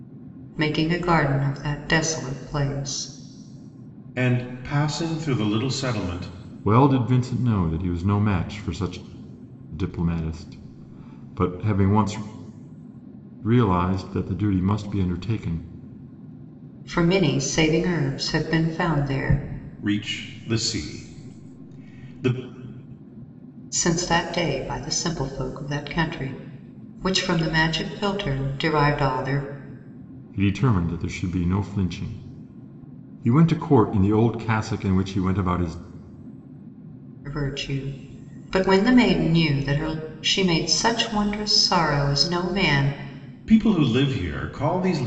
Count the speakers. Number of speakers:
three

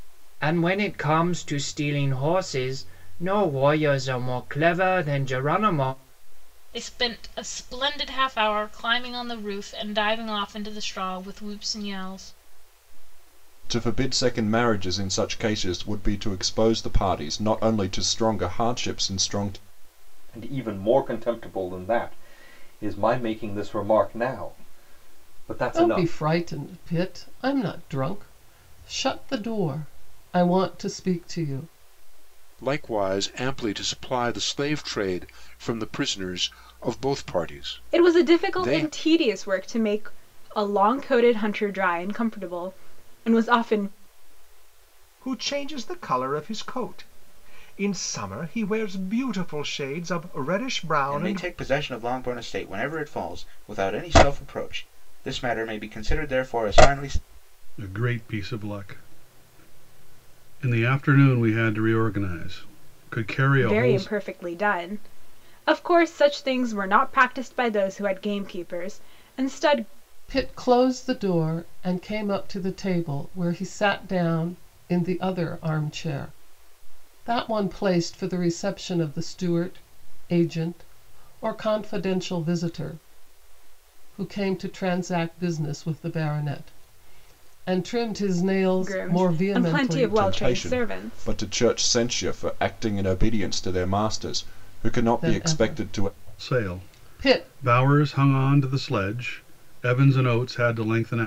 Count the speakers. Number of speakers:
ten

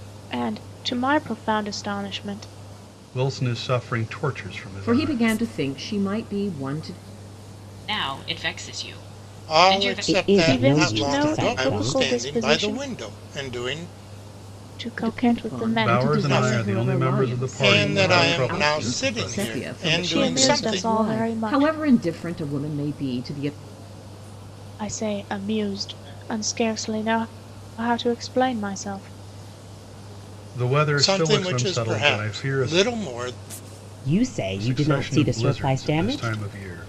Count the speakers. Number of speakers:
six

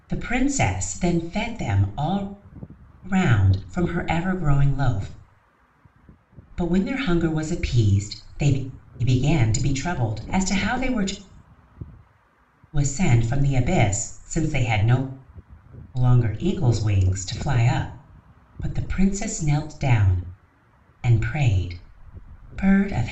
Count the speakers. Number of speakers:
one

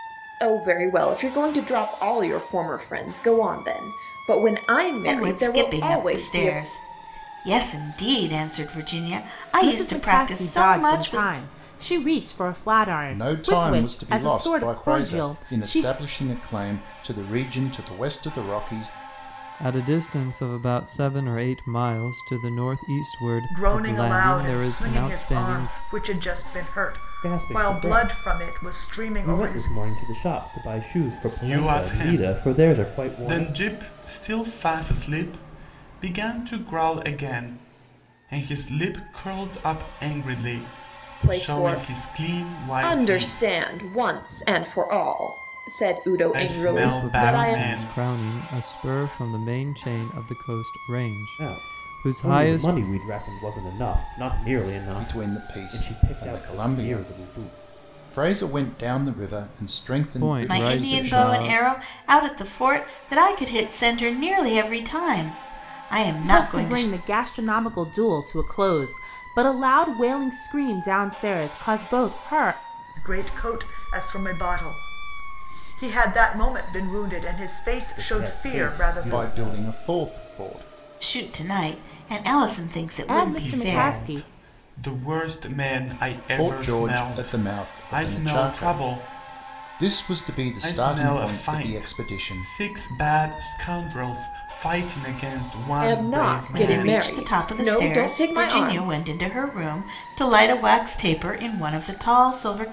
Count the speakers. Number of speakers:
eight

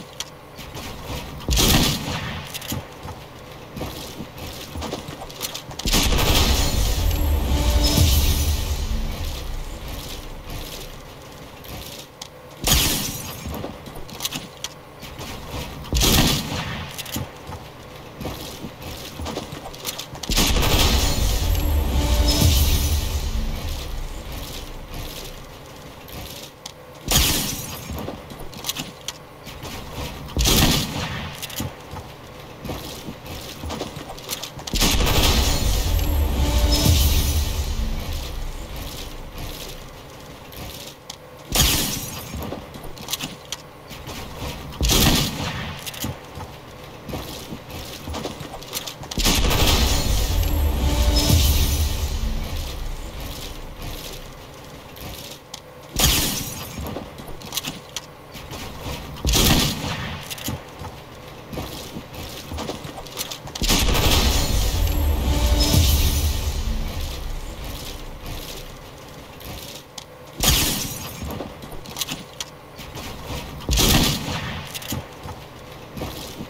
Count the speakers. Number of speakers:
zero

